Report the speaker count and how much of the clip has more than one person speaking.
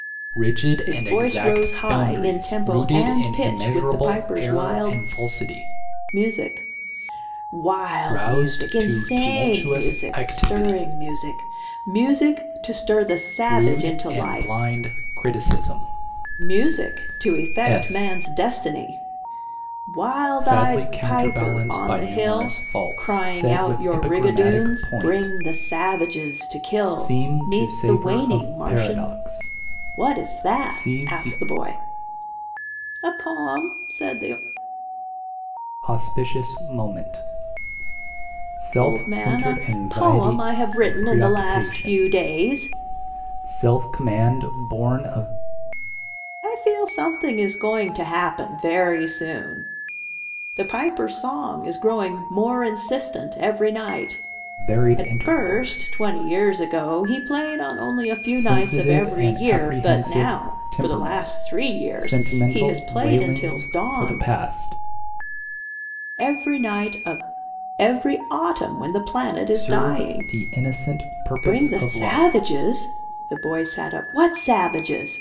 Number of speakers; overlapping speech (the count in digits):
2, about 41%